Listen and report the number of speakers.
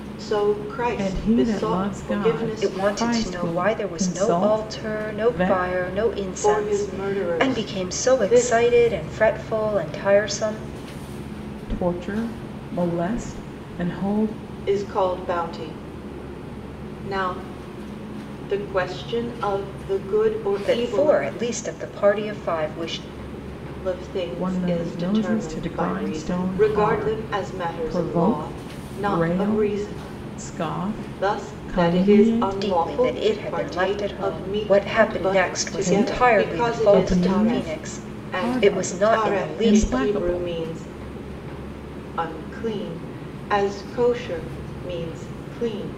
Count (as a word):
three